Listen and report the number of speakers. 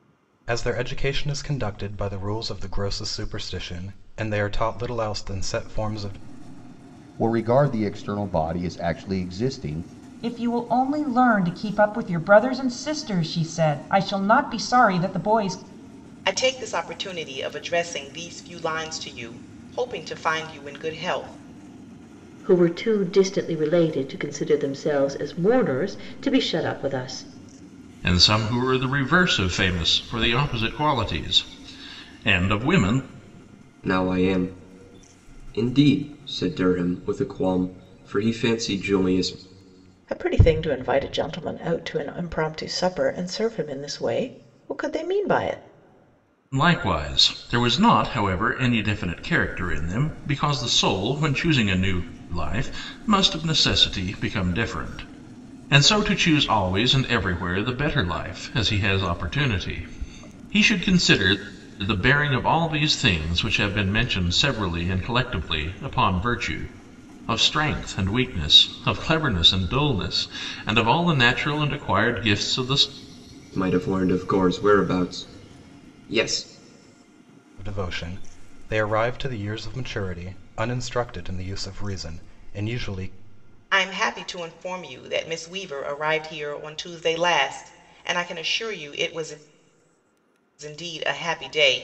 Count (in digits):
8